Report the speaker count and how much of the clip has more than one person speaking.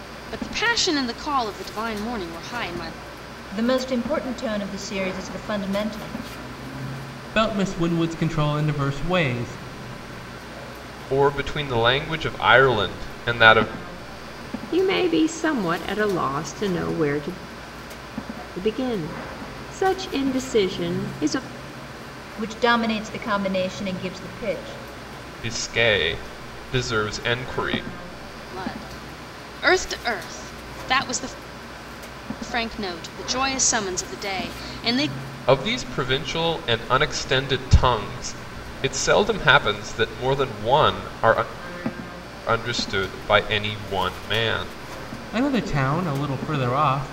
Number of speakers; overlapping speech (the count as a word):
five, no overlap